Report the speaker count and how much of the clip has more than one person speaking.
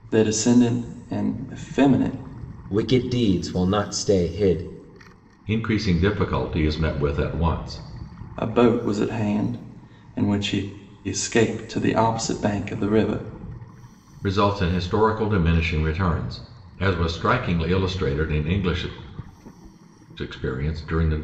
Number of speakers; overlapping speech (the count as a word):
three, no overlap